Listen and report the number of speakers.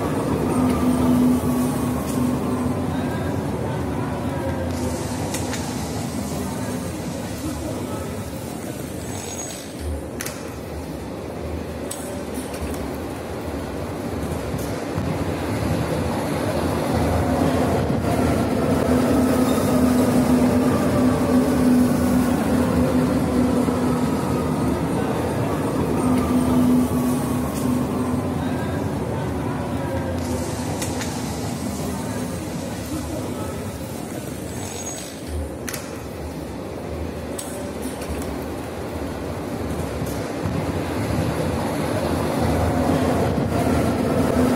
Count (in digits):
0